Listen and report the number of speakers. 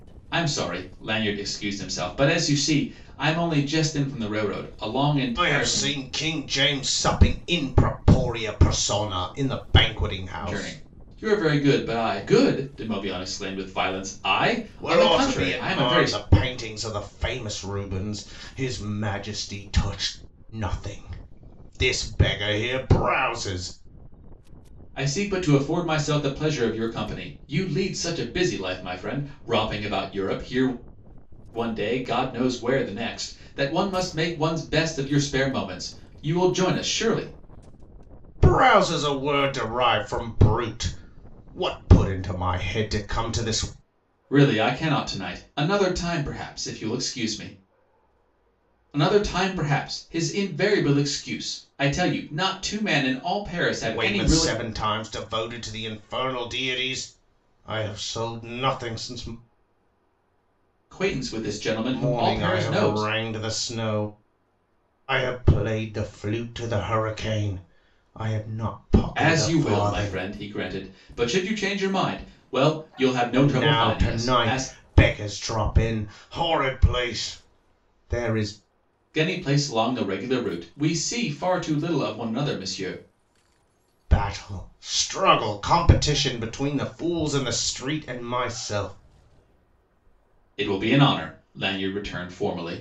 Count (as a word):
two